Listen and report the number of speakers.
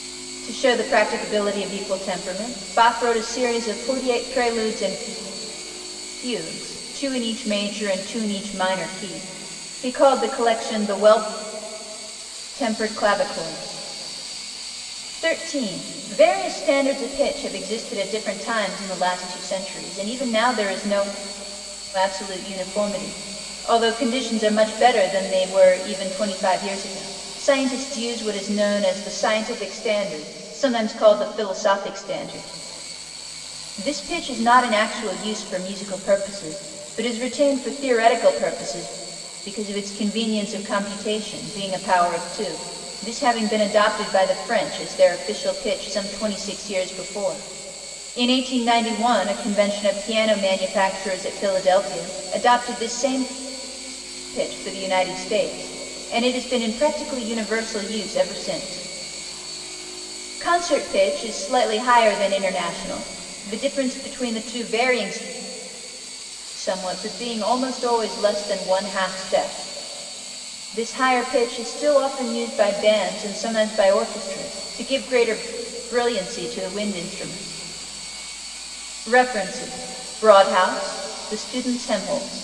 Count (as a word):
one